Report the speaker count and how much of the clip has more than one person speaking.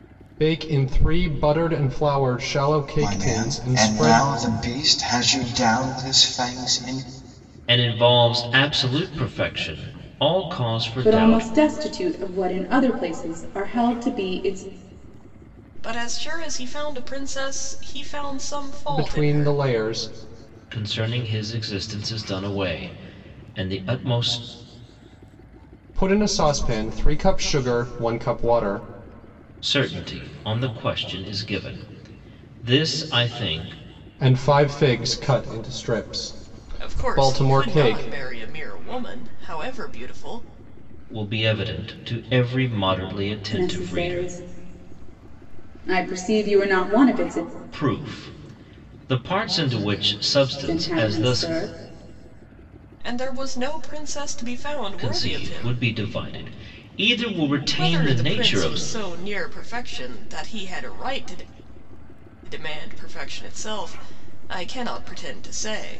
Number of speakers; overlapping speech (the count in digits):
5, about 12%